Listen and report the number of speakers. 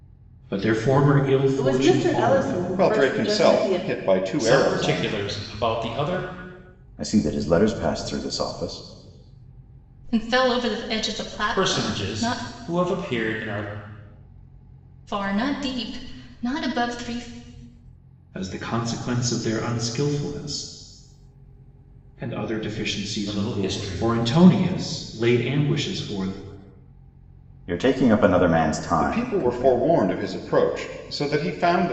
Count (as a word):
six